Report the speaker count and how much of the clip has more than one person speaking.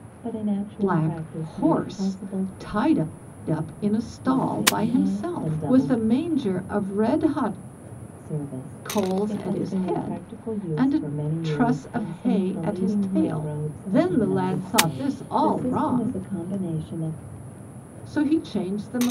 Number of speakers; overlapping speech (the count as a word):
two, about 55%